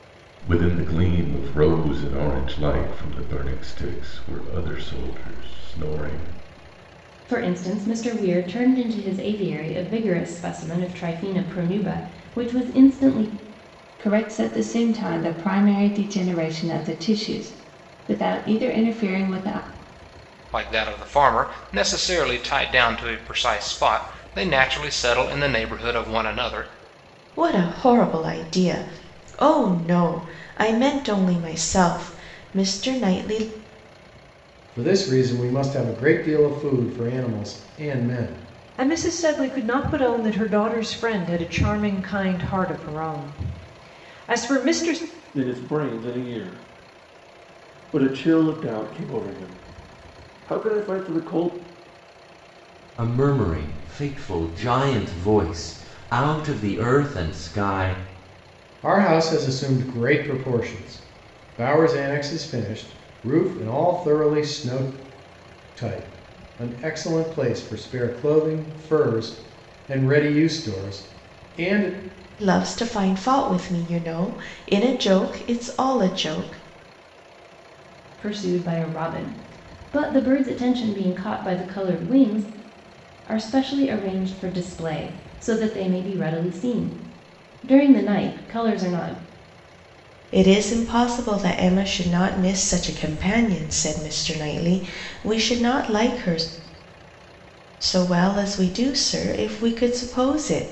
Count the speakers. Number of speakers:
9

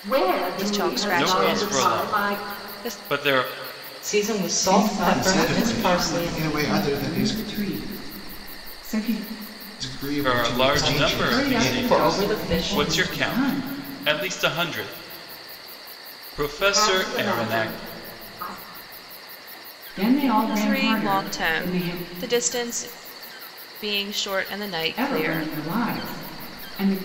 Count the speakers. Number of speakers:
6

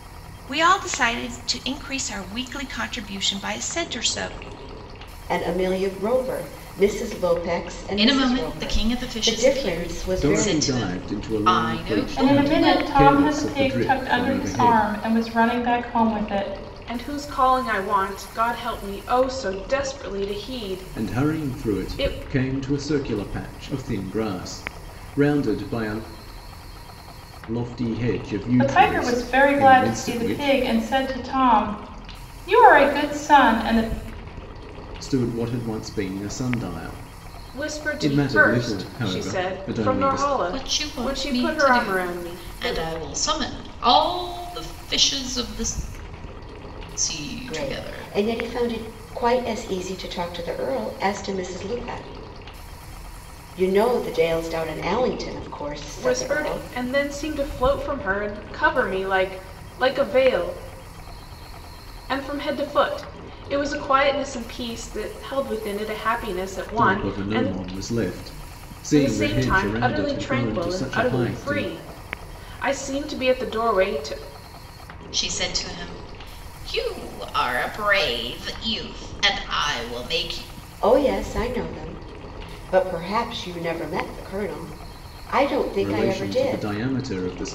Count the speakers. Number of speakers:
6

